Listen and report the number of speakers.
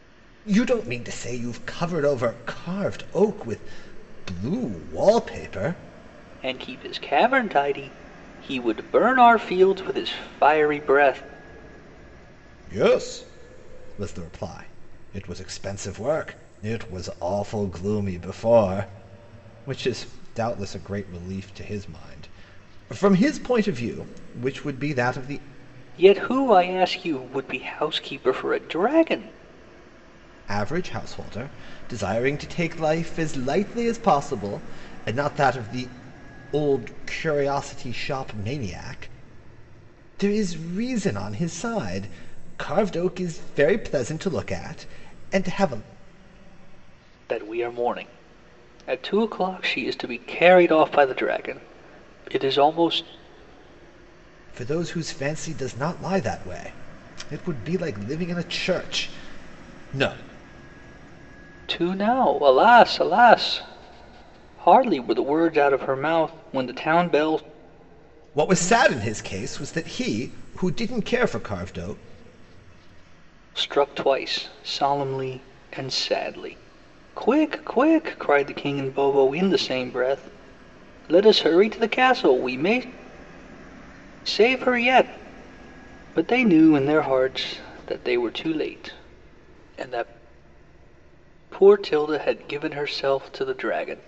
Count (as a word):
two